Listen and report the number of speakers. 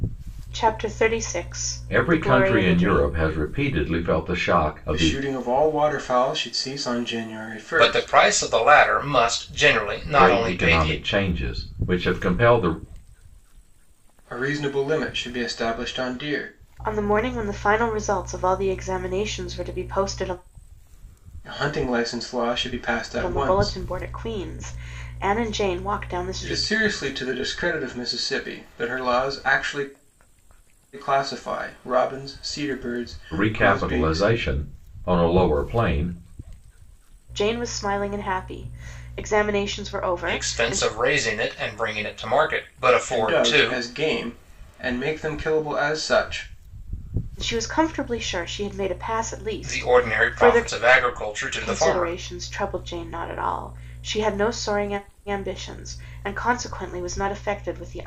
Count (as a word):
four